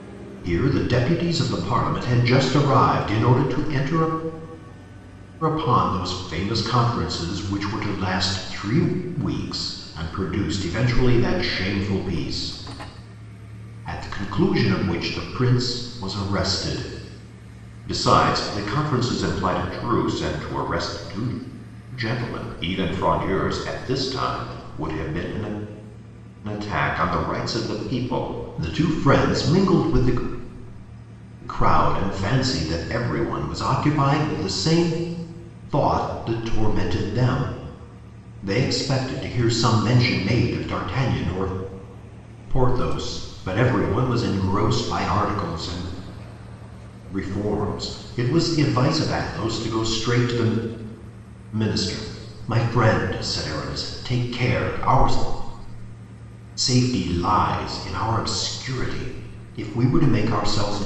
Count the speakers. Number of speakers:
1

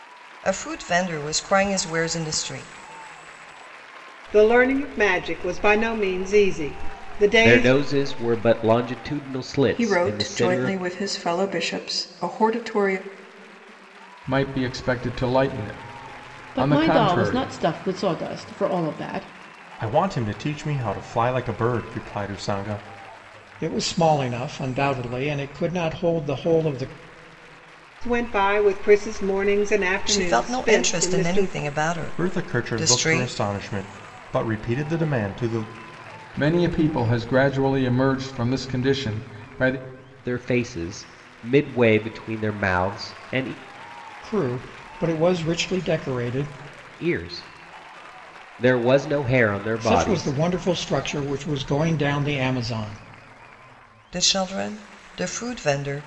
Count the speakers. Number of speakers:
8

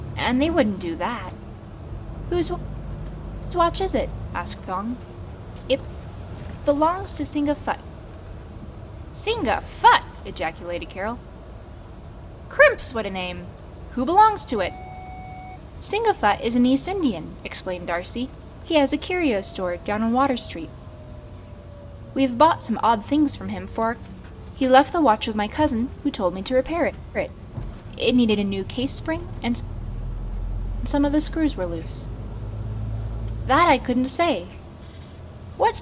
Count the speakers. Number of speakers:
1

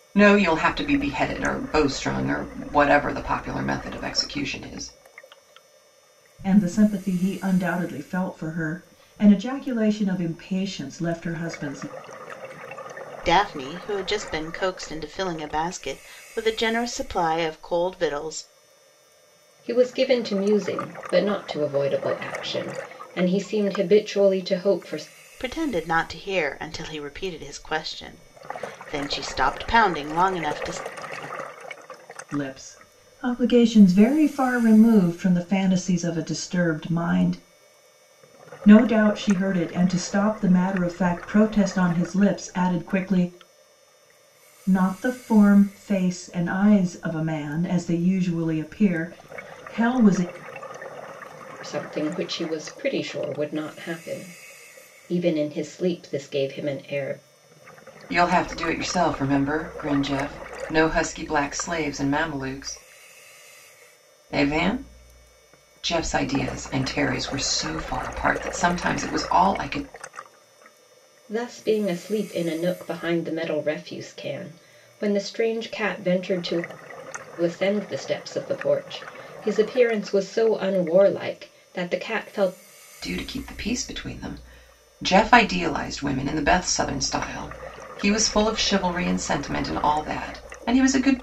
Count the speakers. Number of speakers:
4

